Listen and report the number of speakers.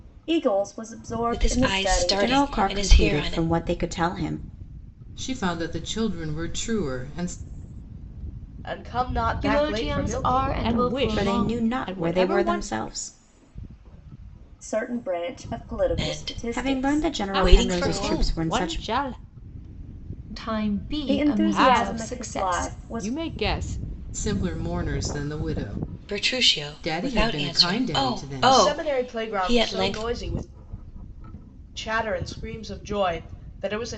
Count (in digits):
7